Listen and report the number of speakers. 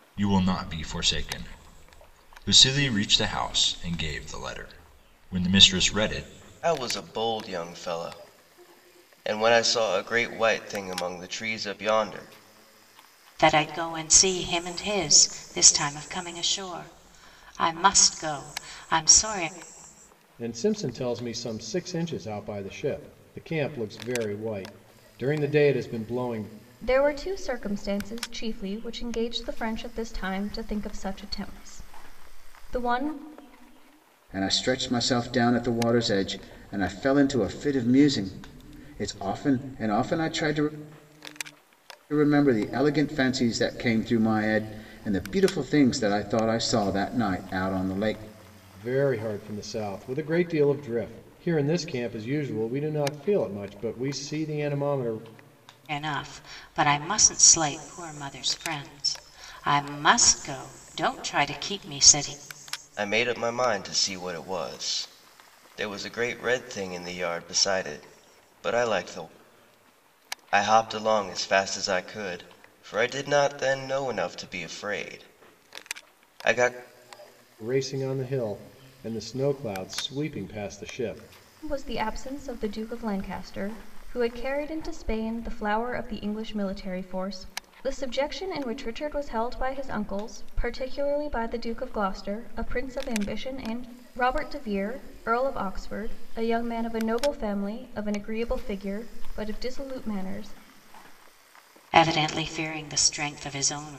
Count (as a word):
six